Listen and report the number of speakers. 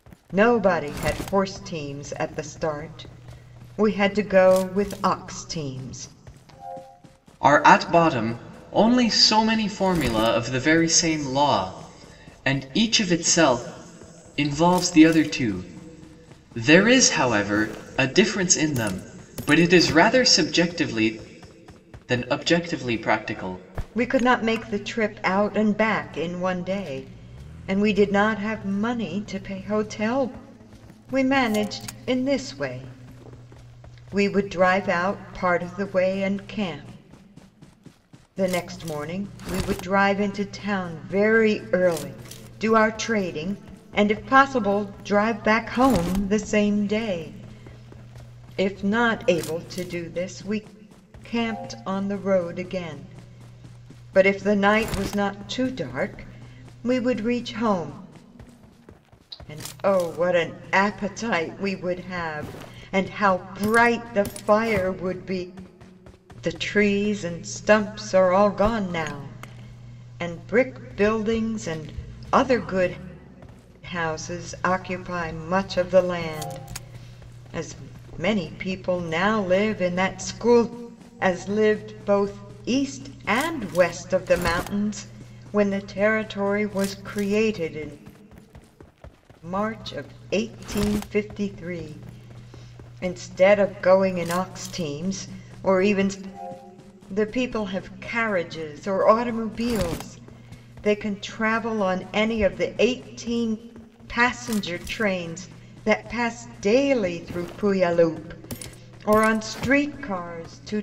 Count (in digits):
2